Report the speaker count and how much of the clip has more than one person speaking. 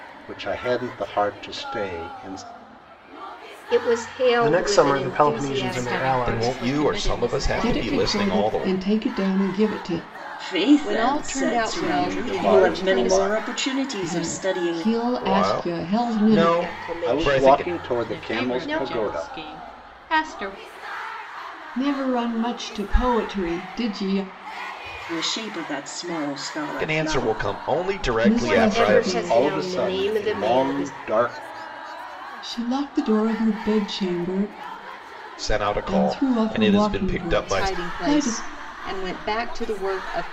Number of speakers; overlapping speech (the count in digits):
8, about 45%